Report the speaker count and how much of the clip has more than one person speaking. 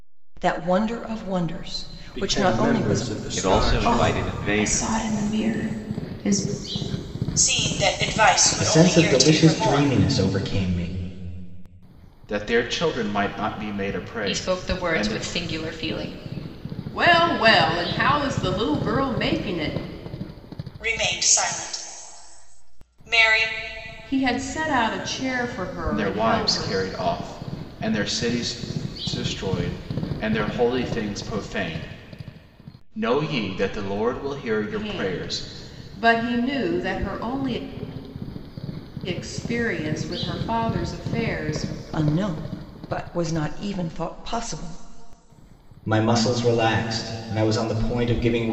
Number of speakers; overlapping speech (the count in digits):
9, about 14%